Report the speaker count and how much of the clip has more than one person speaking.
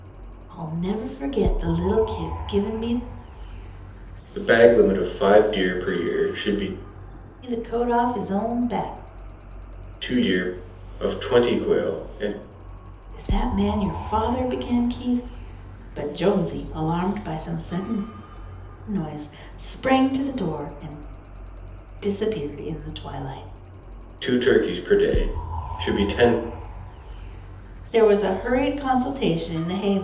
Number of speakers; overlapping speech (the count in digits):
2, no overlap